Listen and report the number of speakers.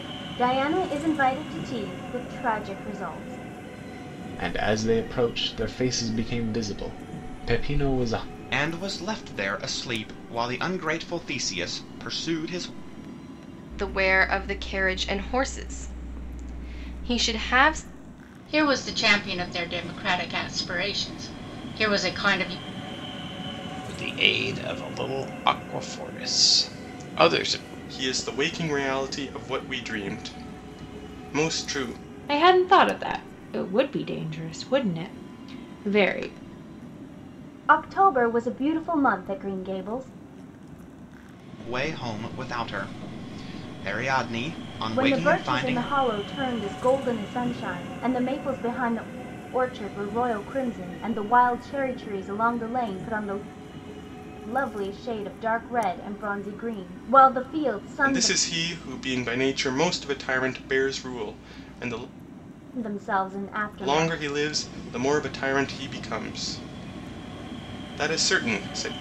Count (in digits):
8